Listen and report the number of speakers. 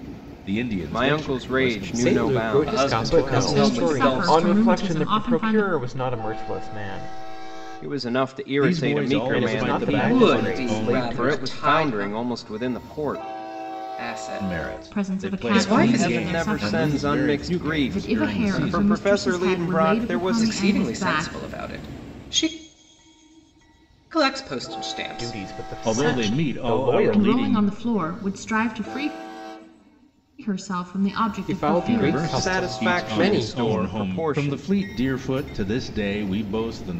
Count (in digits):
6